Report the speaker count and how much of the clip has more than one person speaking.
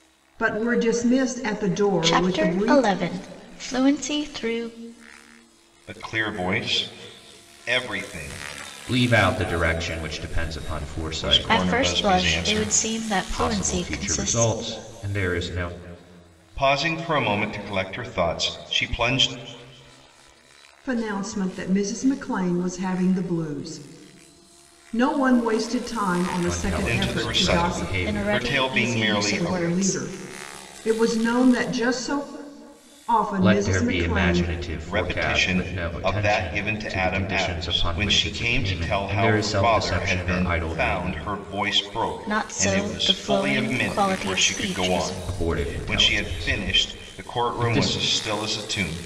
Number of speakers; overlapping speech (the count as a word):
four, about 42%